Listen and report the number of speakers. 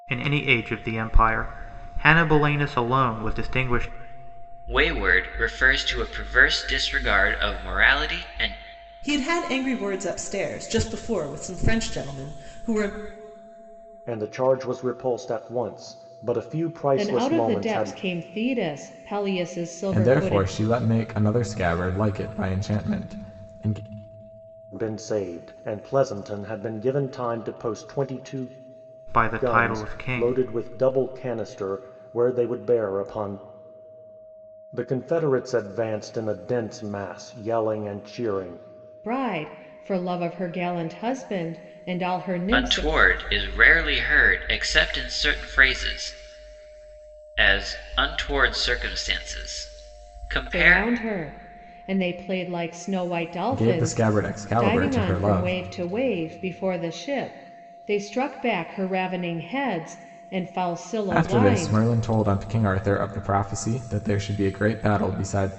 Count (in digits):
6